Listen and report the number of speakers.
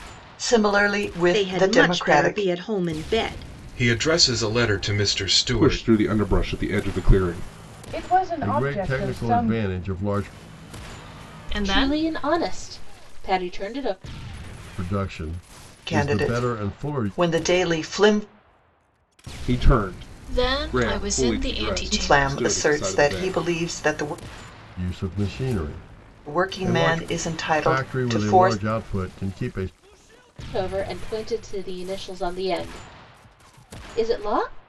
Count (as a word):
eight